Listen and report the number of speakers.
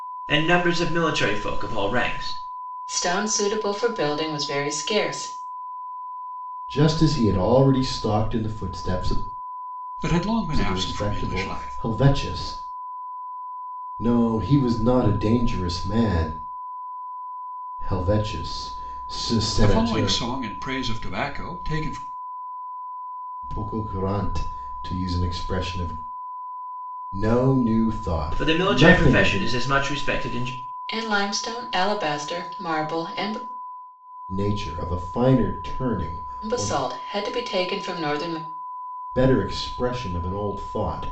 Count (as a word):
four